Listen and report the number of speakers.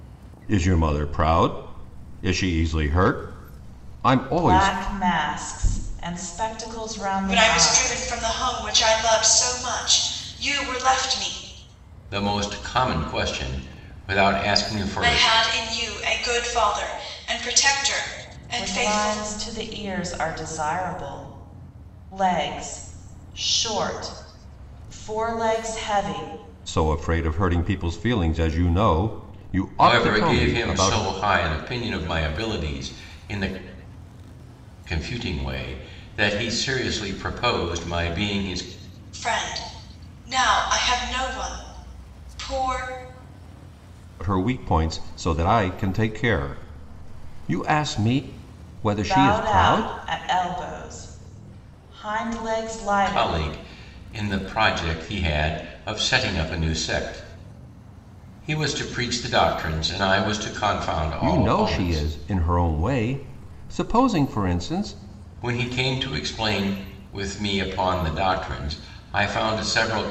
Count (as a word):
four